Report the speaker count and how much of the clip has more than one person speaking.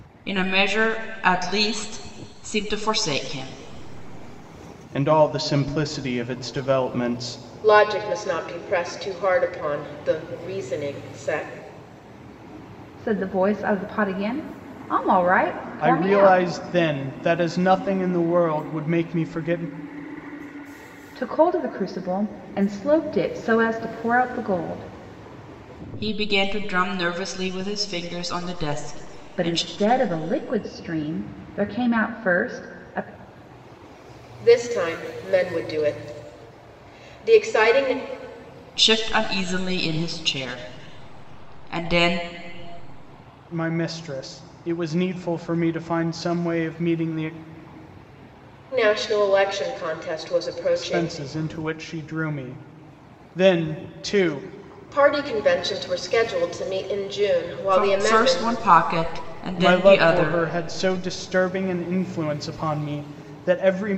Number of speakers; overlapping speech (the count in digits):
4, about 5%